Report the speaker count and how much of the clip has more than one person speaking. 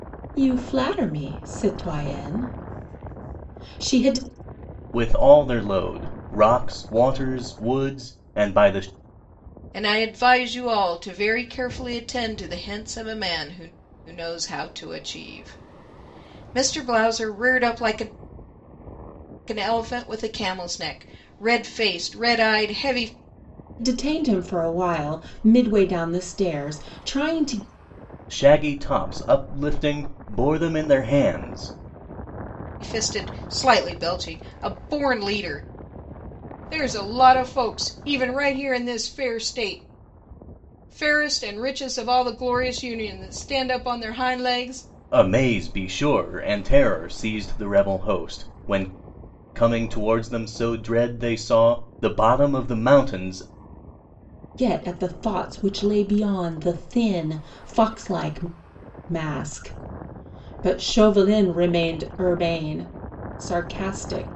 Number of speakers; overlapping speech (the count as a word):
three, no overlap